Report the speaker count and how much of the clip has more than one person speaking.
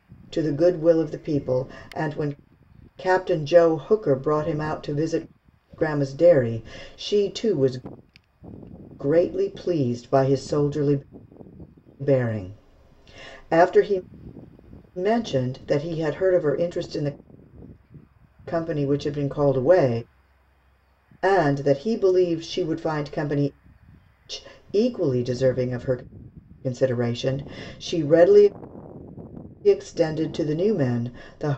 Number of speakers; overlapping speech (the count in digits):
1, no overlap